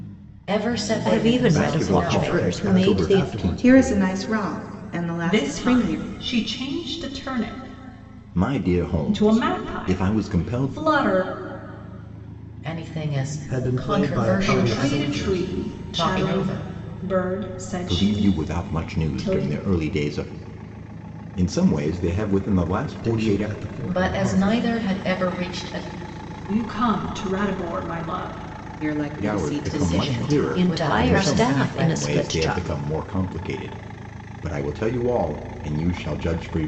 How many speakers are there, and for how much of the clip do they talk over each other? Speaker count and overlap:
6, about 41%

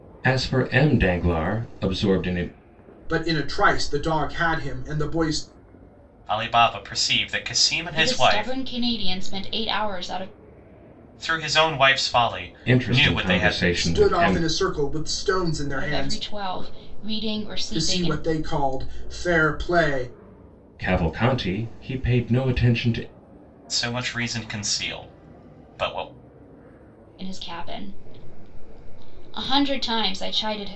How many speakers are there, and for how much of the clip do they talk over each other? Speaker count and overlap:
4, about 11%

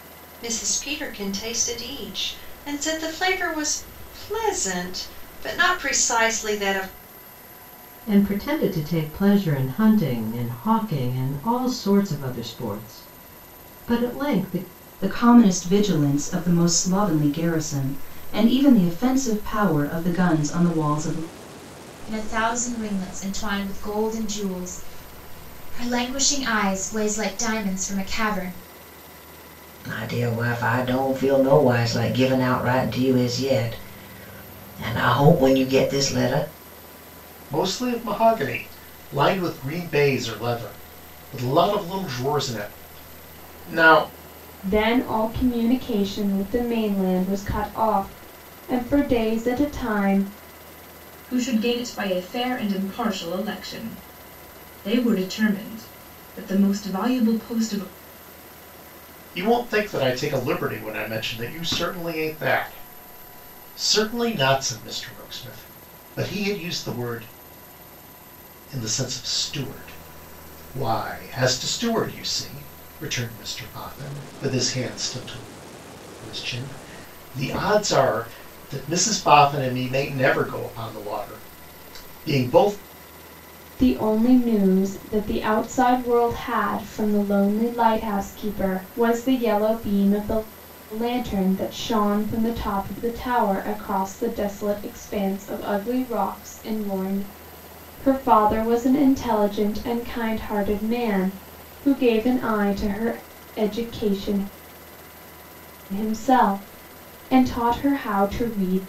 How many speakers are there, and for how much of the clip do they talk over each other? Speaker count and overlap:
8, no overlap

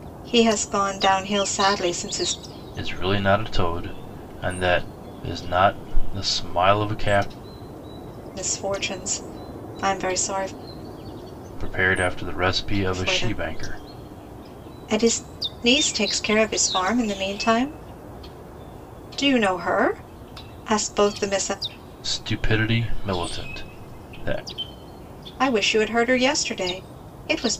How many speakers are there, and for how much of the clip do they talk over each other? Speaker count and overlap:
2, about 3%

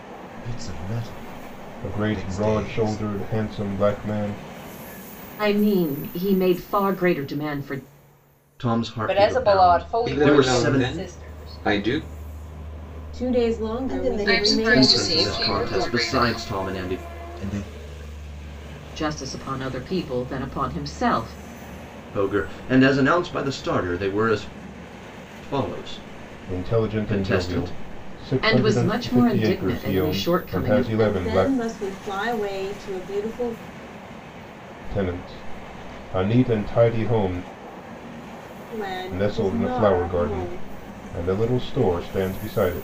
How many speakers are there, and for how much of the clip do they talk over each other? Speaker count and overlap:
9, about 31%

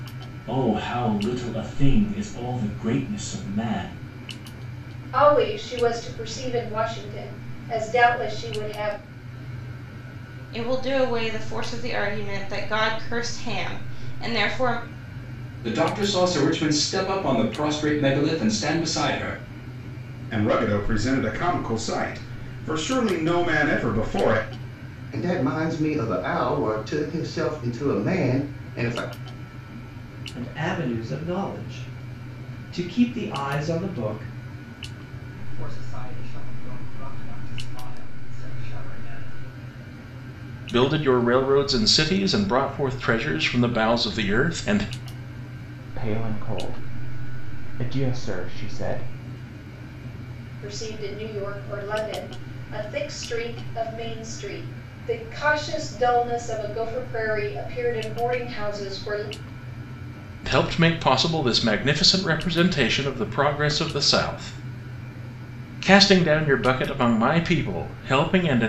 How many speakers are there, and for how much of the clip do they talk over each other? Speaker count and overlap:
10, no overlap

